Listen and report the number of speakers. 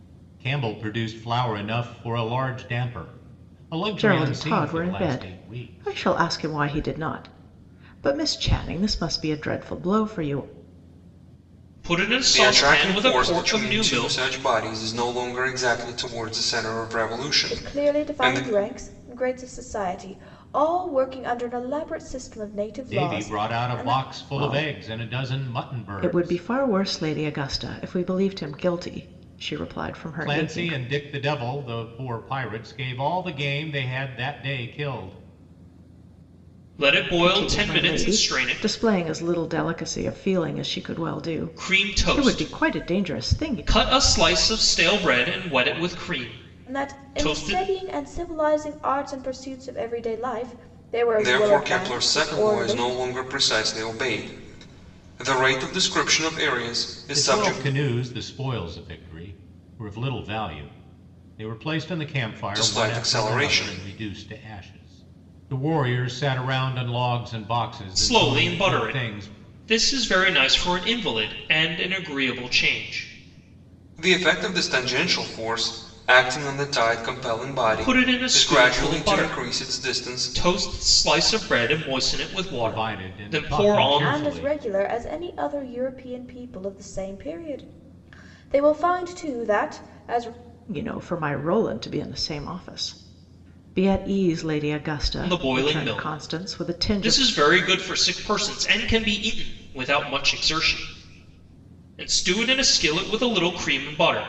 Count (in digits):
5